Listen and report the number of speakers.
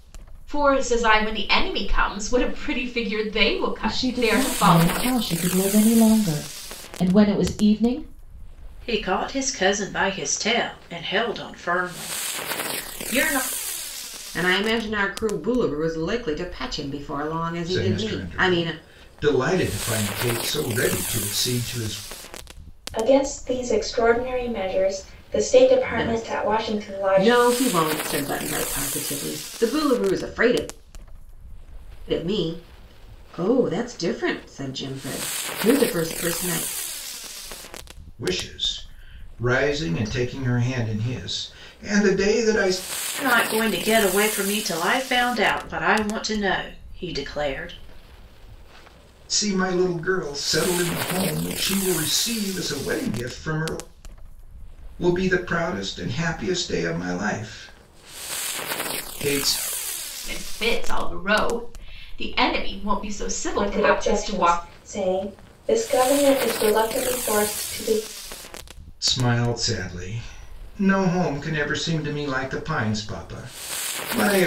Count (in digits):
6